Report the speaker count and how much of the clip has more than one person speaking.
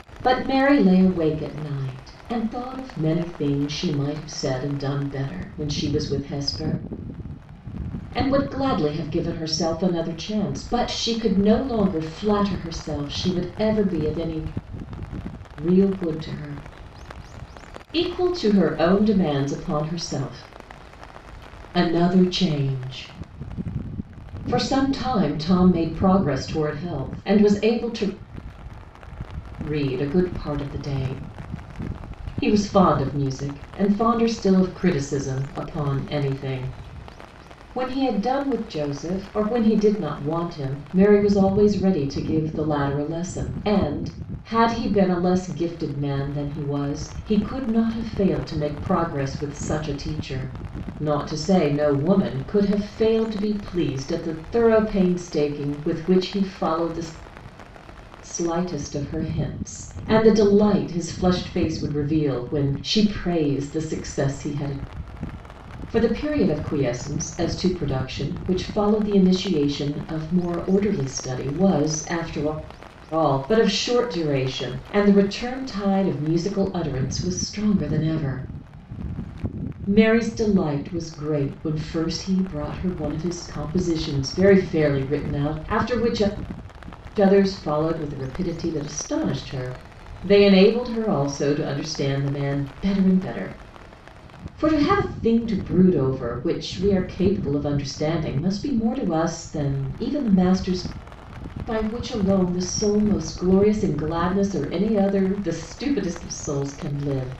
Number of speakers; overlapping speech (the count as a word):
one, no overlap